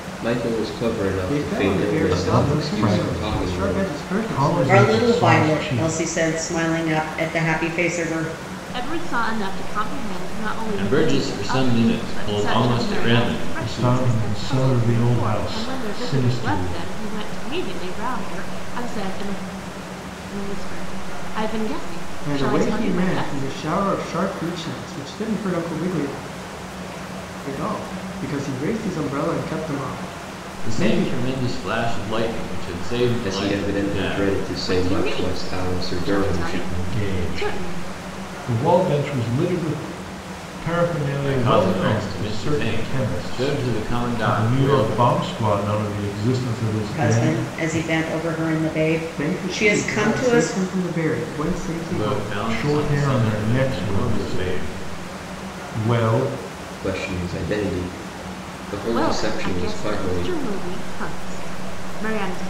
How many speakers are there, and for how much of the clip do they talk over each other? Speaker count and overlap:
six, about 43%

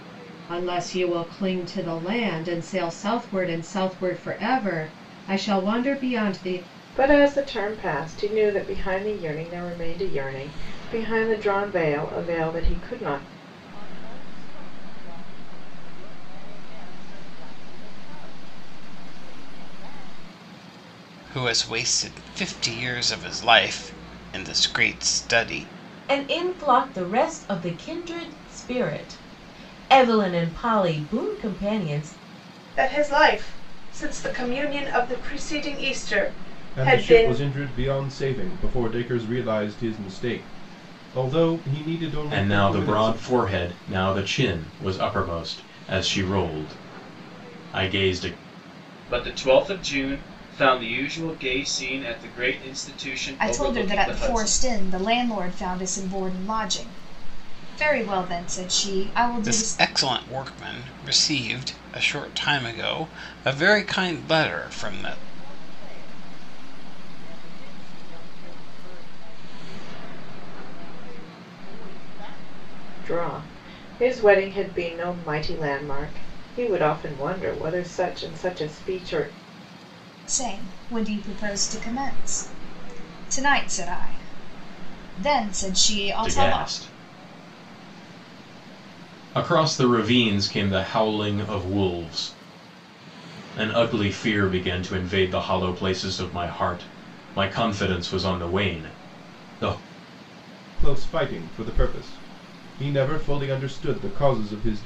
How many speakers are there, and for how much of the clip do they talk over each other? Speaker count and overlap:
ten, about 4%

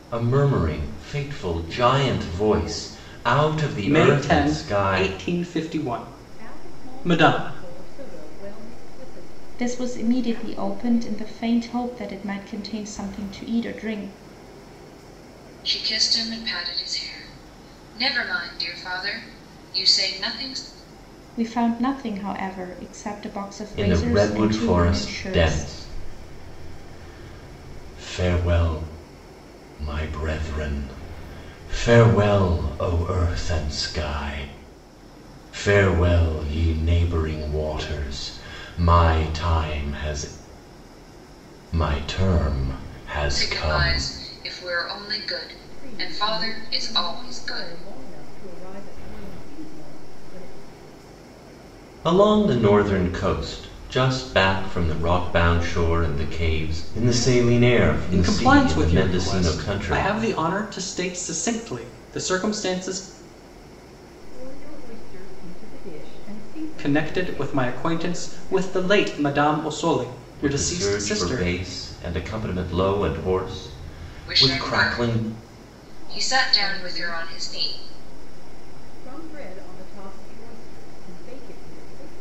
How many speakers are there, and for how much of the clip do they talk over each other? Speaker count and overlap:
five, about 26%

